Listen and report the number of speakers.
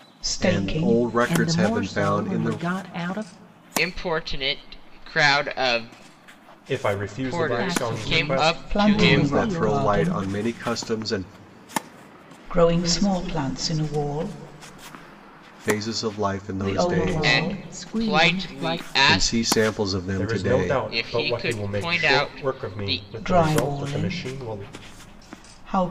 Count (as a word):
five